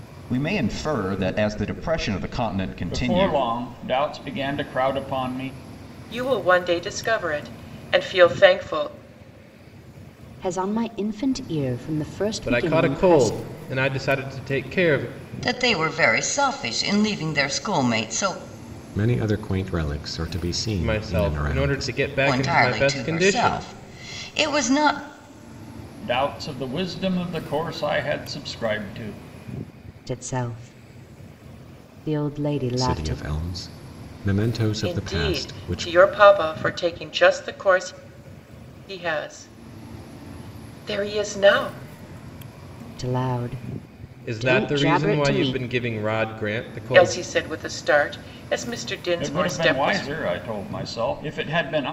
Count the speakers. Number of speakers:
7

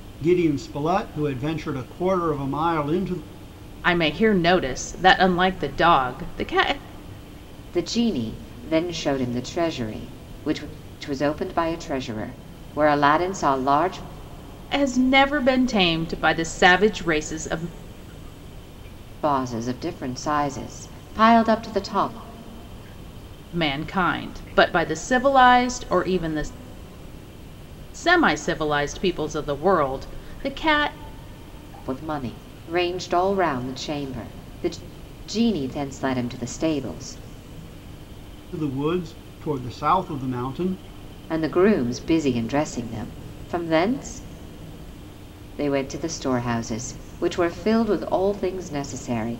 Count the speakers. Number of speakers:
3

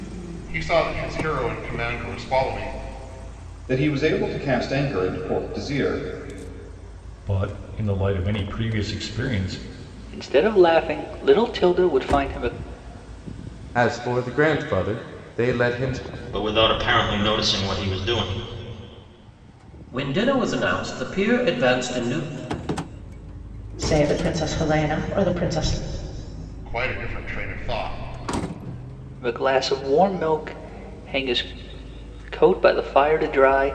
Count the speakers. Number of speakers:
8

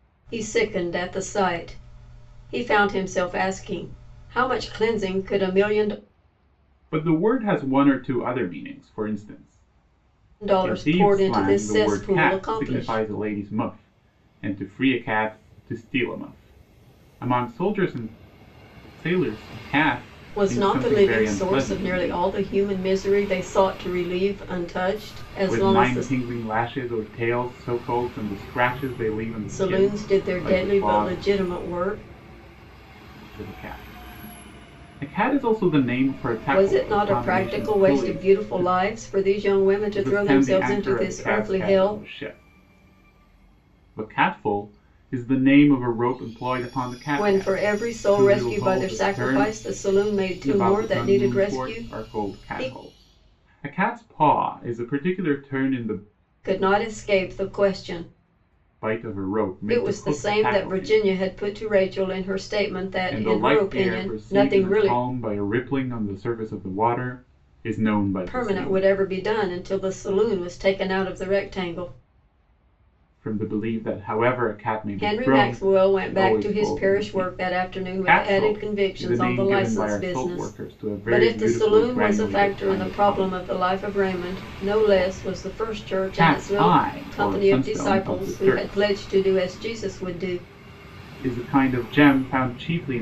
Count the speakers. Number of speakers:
2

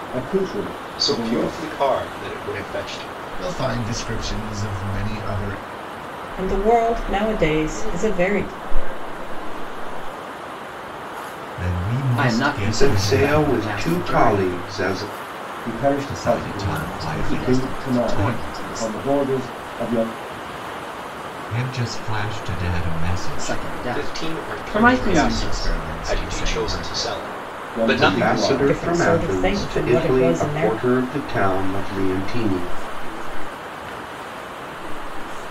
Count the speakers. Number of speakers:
8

